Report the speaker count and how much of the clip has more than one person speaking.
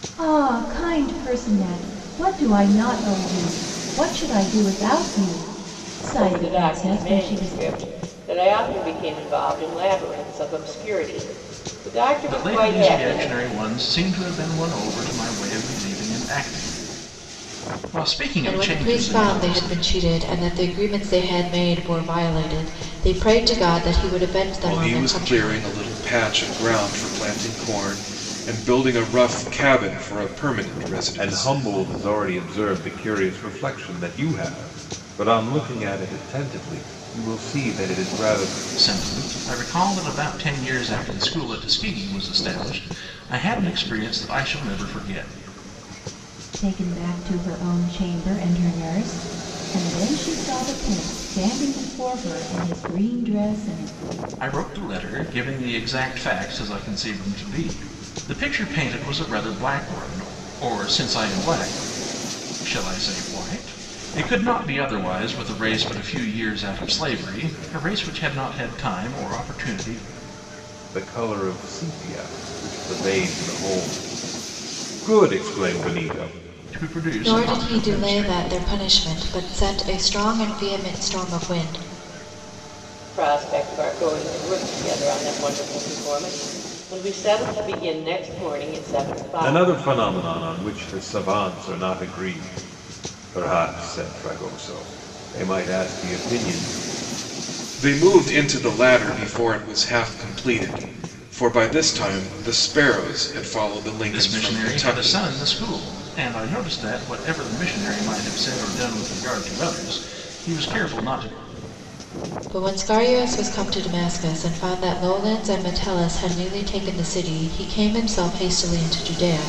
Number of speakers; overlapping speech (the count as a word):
six, about 7%